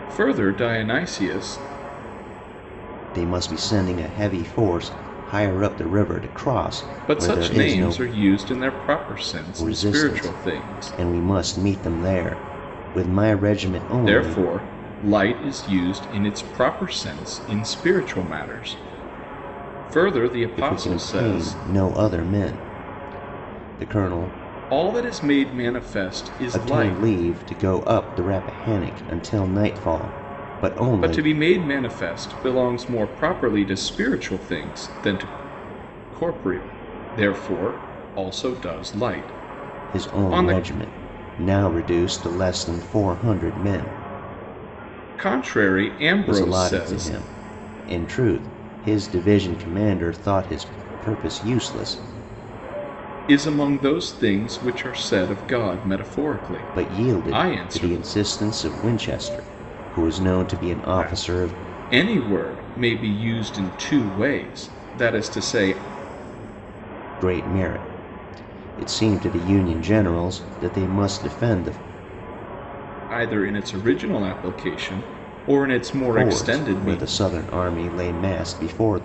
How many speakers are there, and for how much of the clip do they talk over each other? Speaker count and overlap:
2, about 12%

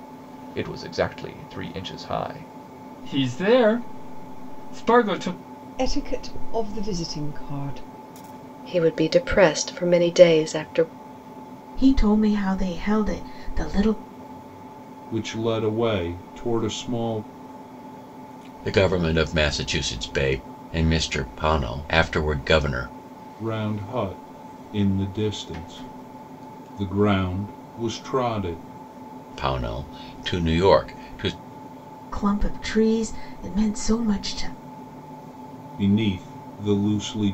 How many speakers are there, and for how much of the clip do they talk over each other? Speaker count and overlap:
7, no overlap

